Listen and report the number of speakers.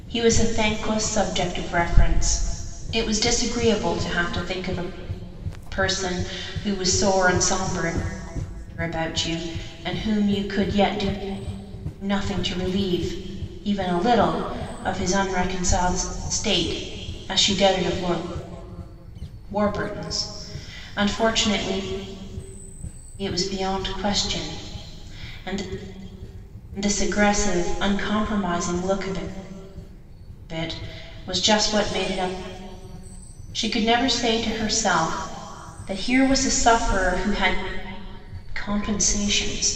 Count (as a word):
one